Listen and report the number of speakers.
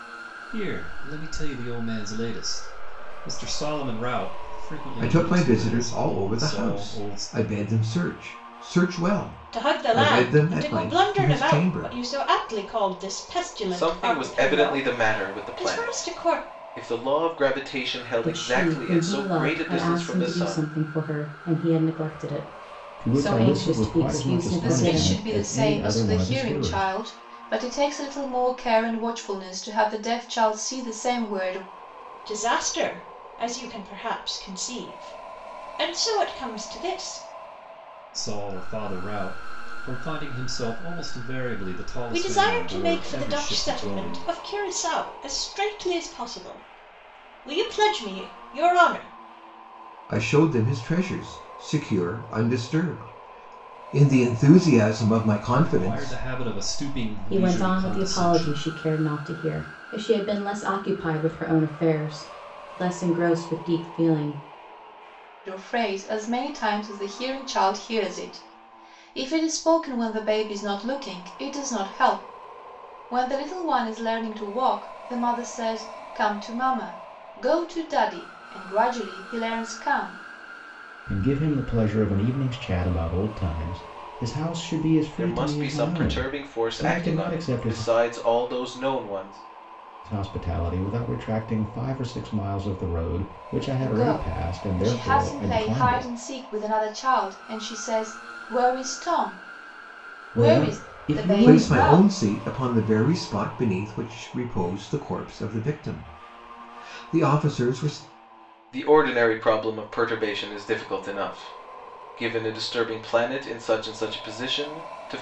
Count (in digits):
7